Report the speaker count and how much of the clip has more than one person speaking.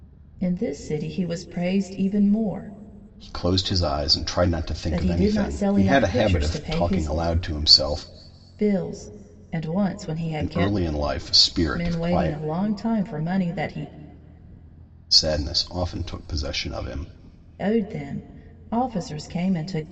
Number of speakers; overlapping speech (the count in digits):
2, about 18%